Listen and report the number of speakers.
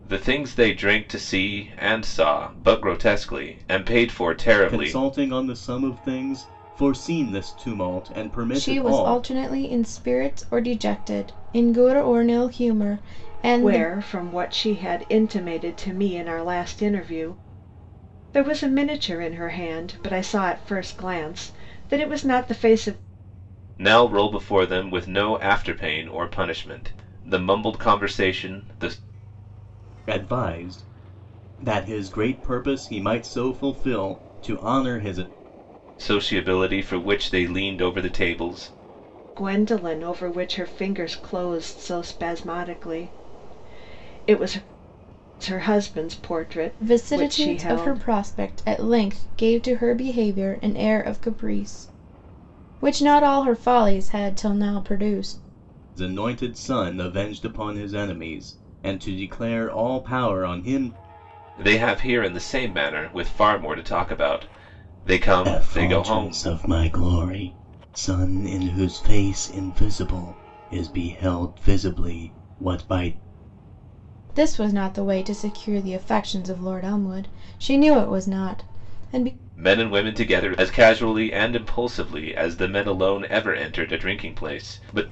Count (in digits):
4